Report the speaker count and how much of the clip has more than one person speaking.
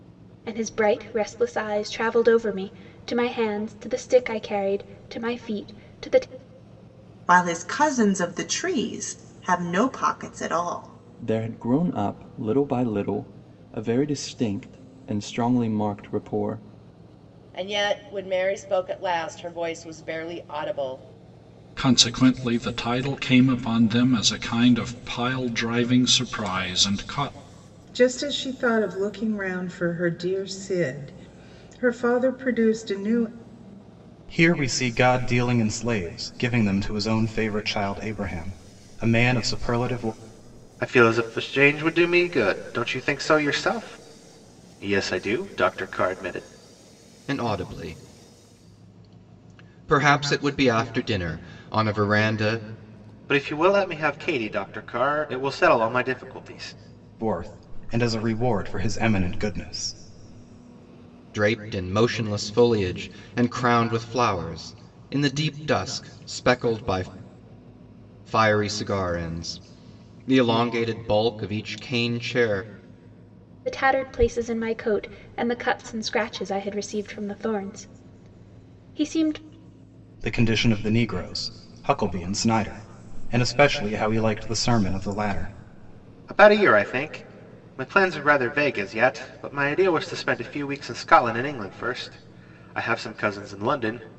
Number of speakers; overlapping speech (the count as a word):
nine, no overlap